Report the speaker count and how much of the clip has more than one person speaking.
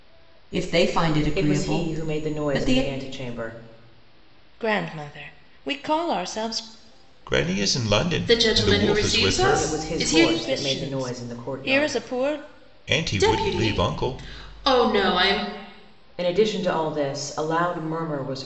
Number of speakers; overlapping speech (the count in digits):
5, about 35%